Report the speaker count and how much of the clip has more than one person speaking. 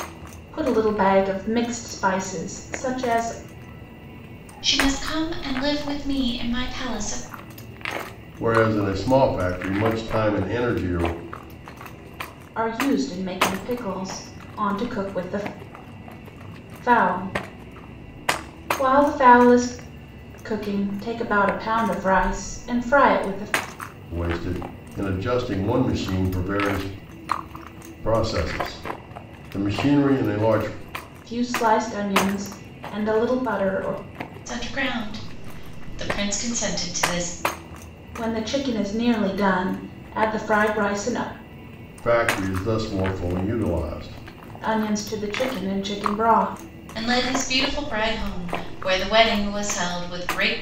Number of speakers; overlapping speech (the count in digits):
3, no overlap